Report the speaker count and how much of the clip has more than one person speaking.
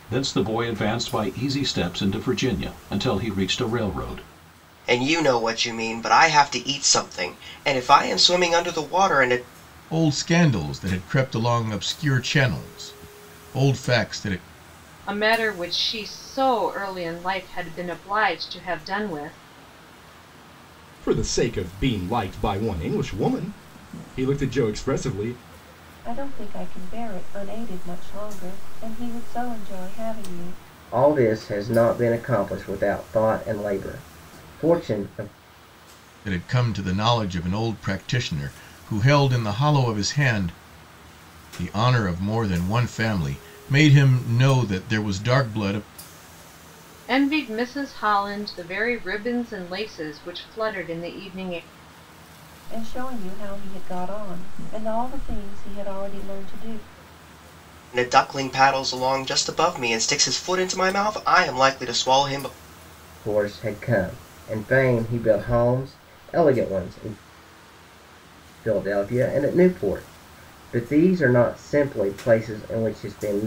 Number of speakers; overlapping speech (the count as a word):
seven, no overlap